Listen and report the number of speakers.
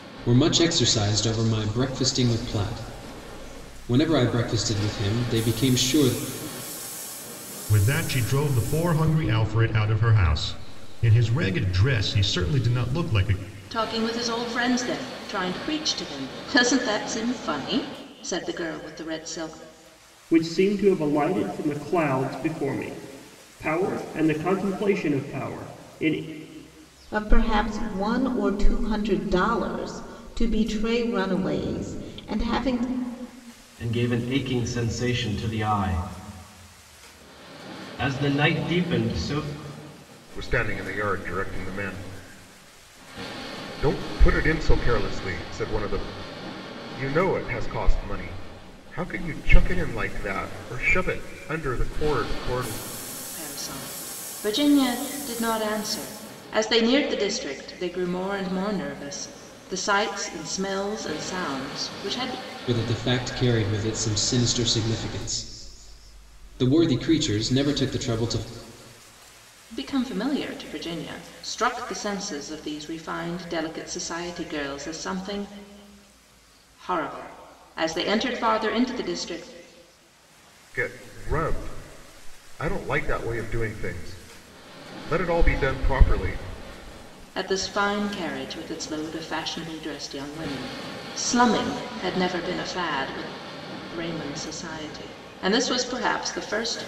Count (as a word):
seven